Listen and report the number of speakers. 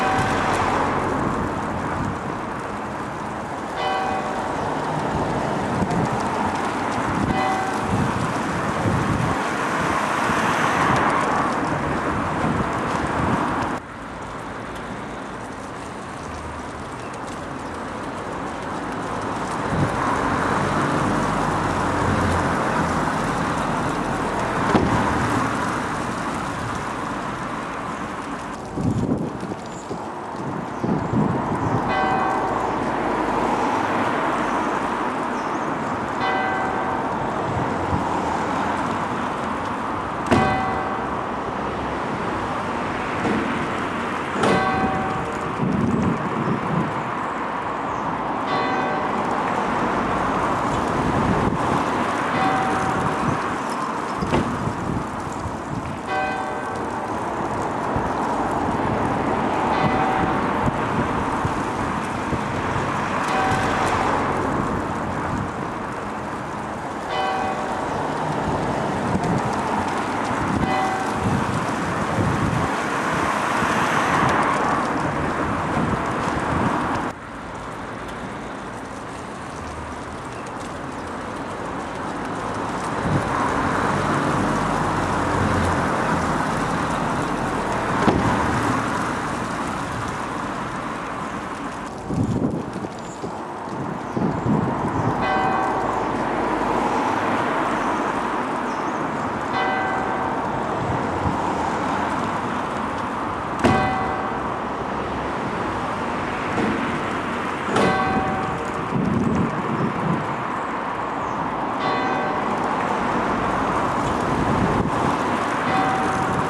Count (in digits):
0